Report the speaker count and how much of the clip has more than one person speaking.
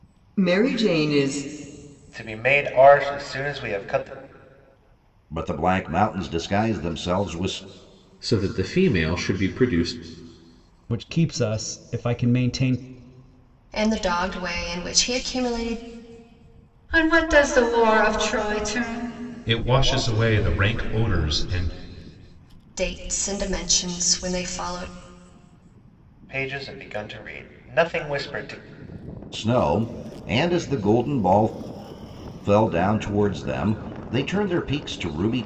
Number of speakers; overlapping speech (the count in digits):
8, no overlap